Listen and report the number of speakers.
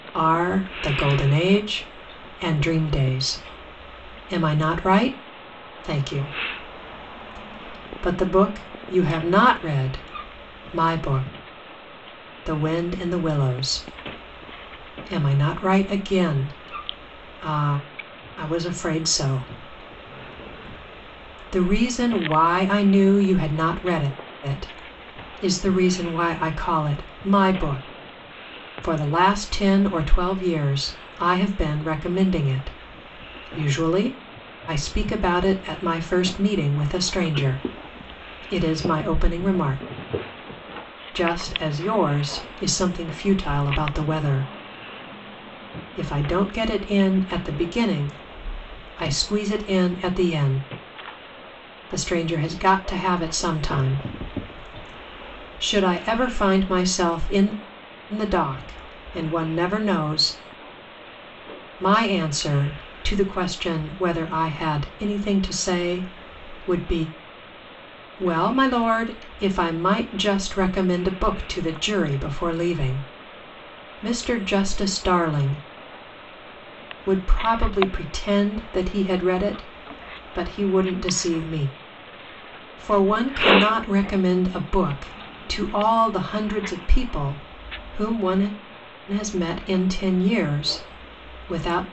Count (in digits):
1